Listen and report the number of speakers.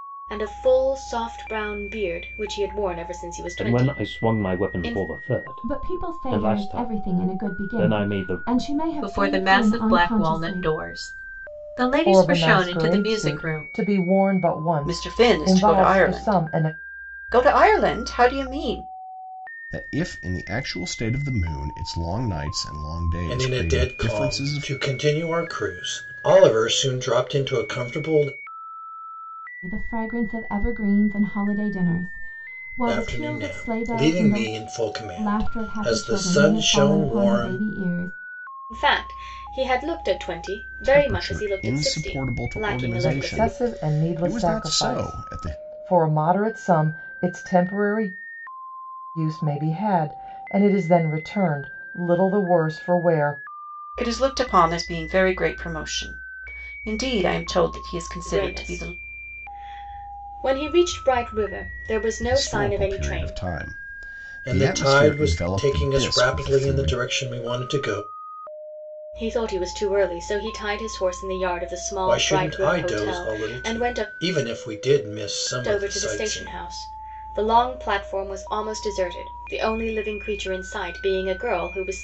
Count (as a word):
eight